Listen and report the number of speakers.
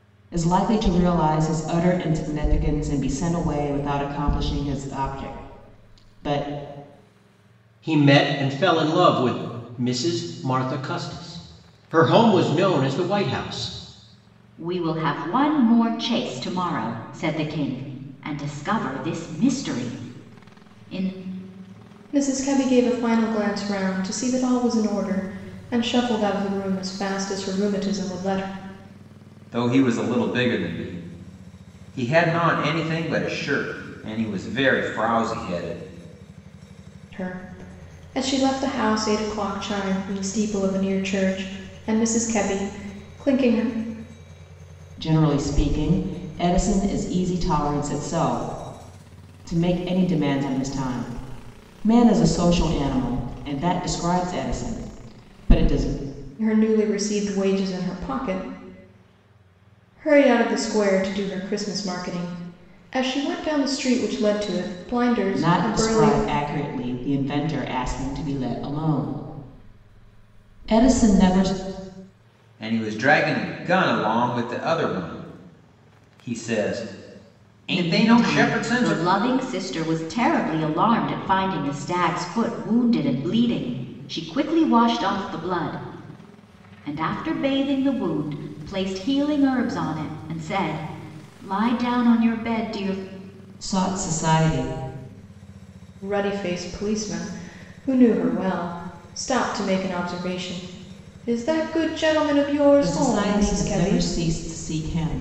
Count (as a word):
five